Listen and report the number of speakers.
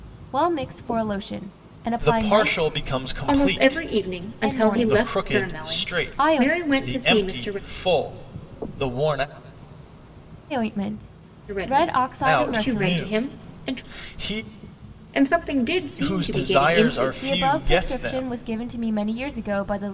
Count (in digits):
3